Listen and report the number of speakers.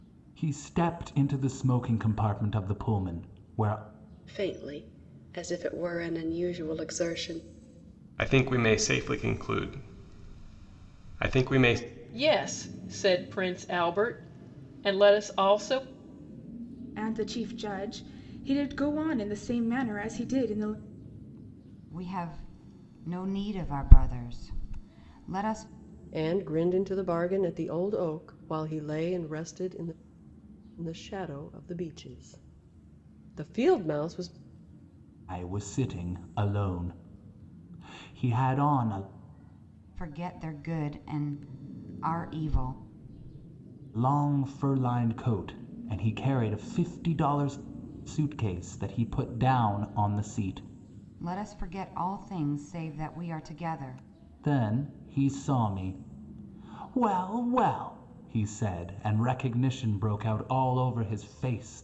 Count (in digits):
7